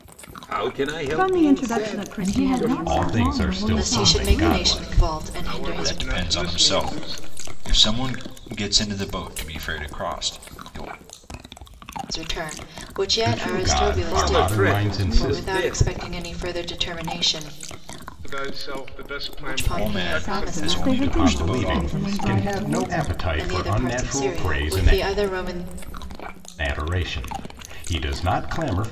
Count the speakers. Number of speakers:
7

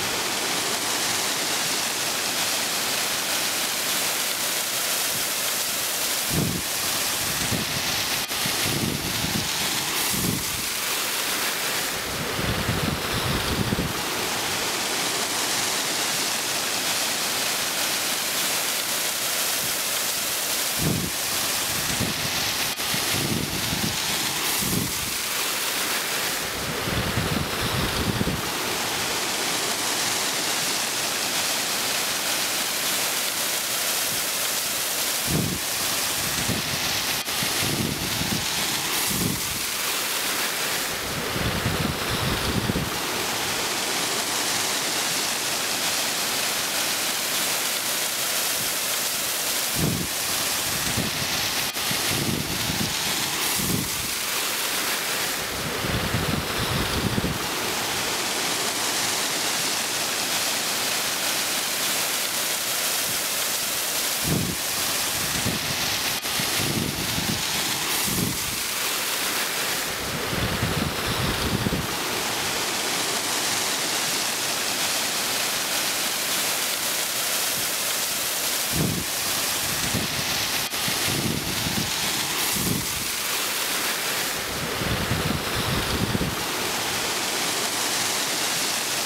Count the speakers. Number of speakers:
0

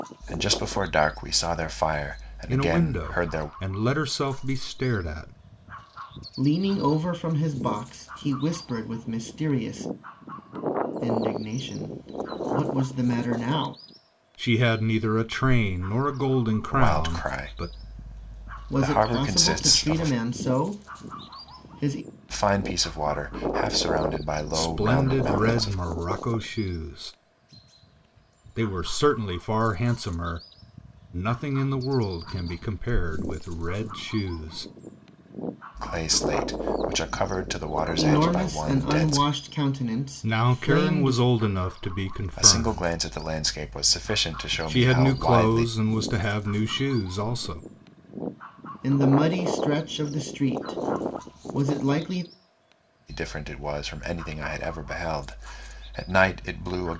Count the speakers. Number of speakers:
3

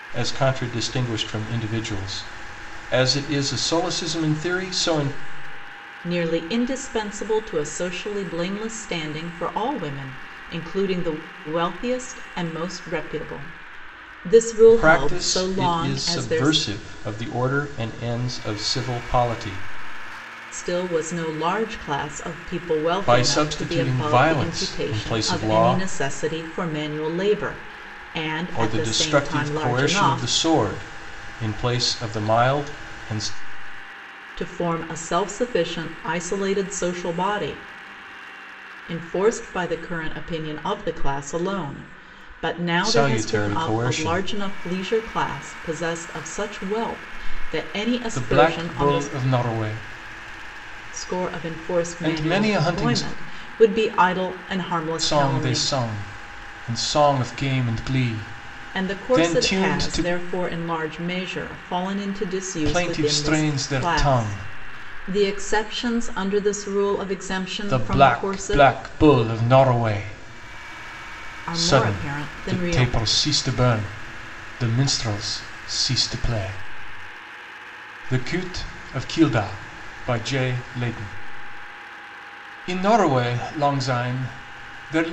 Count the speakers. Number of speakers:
2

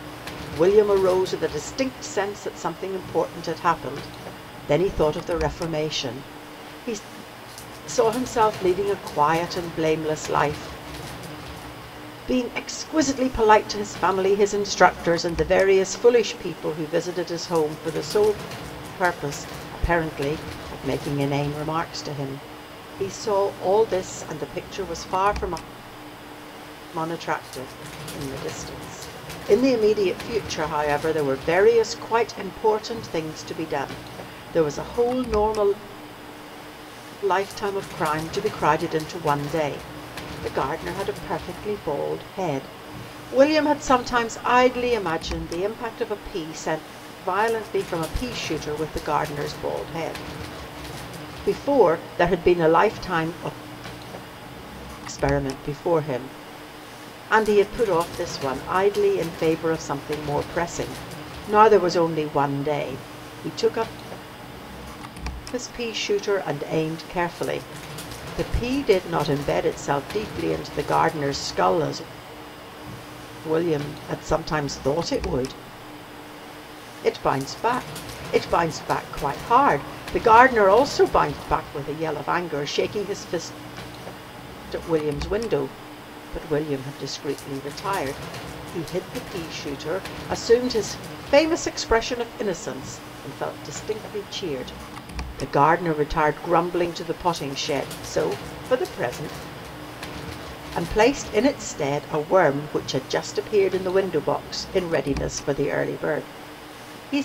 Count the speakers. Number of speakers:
1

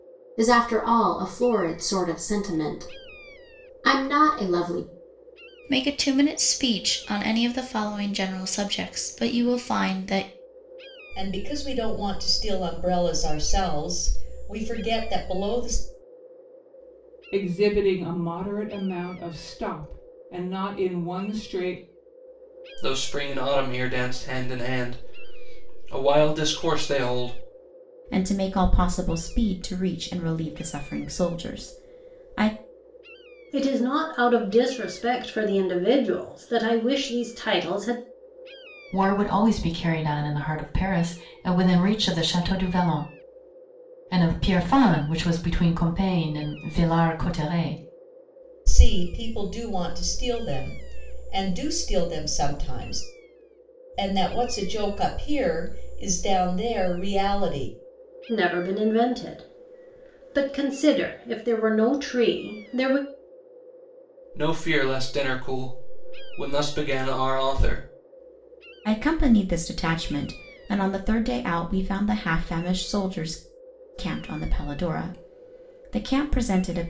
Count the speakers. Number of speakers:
8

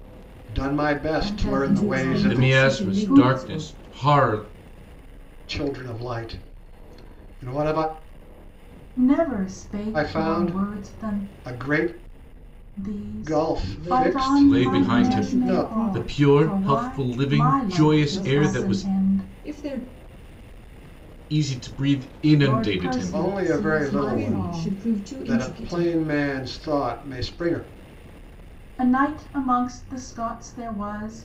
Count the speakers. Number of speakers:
4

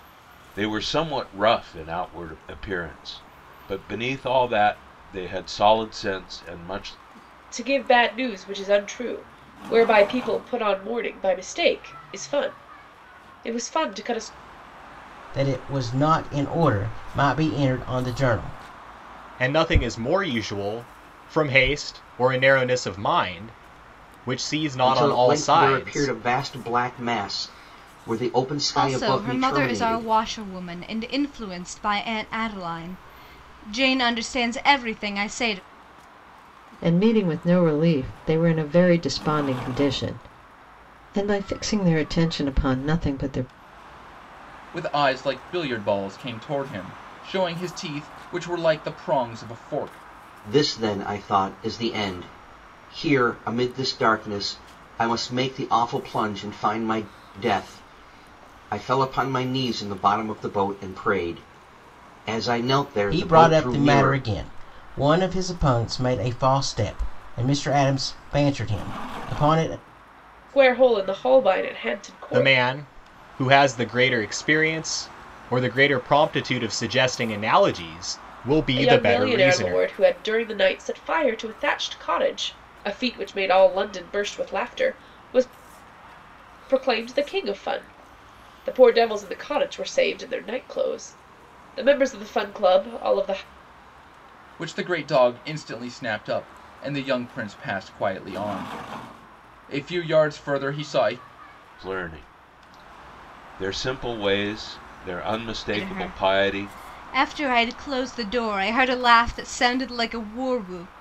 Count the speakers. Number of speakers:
8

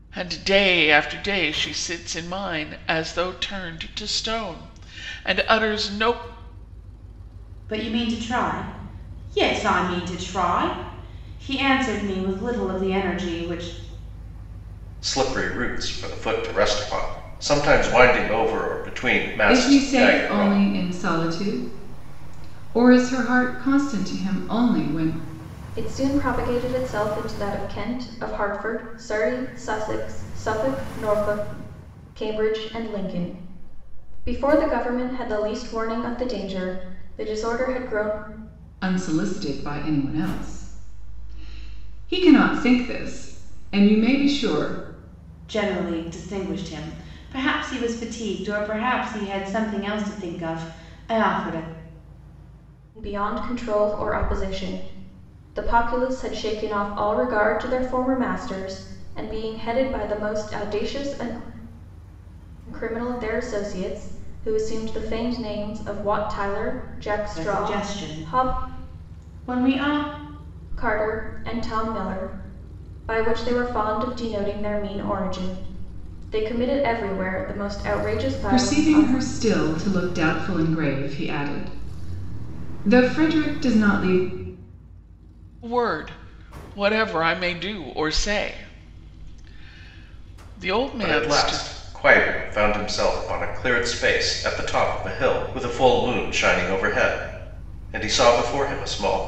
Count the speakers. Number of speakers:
5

